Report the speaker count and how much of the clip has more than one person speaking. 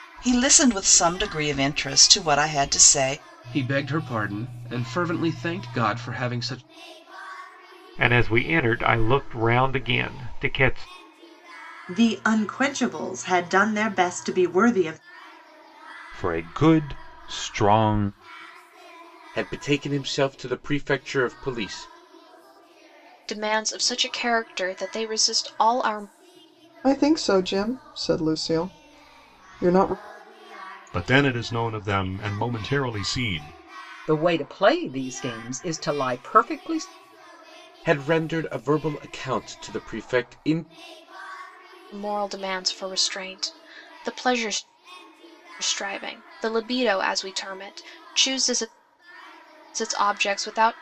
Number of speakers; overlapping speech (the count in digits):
10, no overlap